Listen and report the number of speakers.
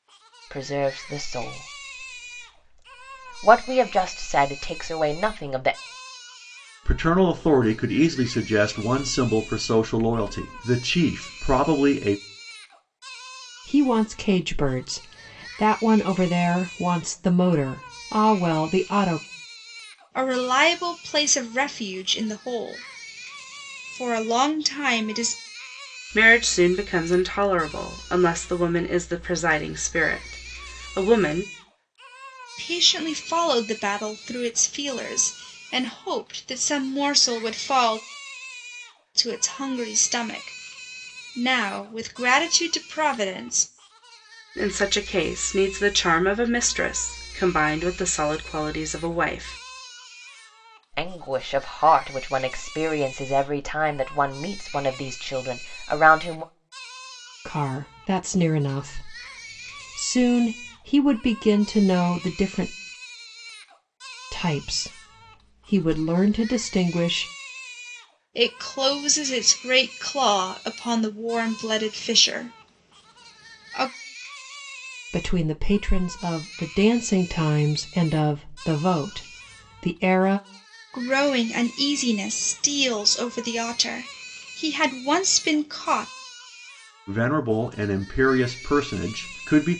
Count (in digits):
5